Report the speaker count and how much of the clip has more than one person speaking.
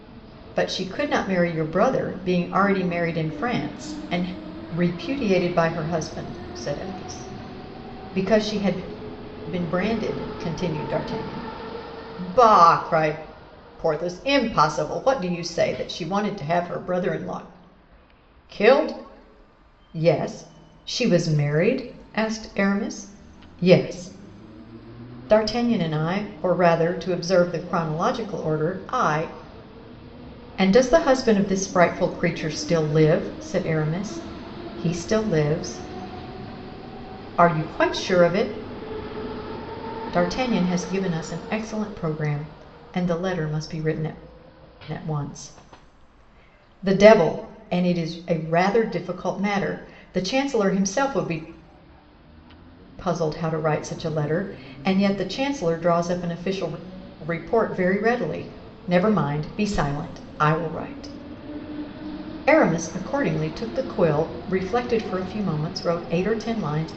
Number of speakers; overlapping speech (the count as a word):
one, no overlap